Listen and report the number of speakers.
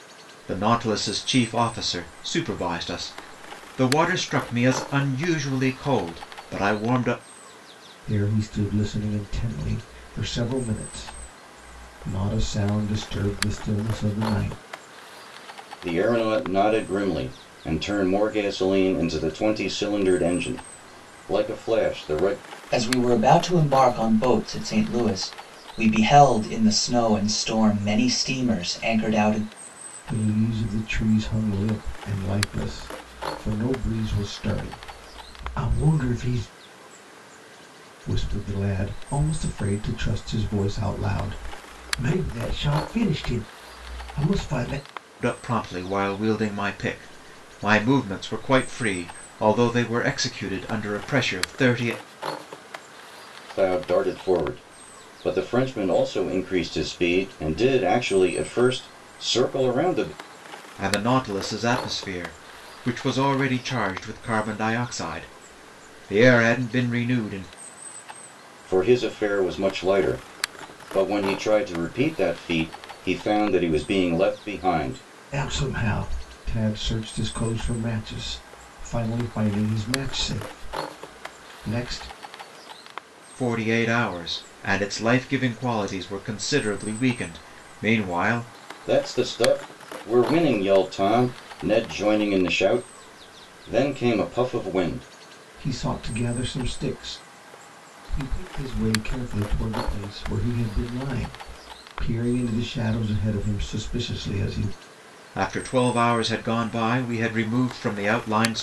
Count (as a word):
four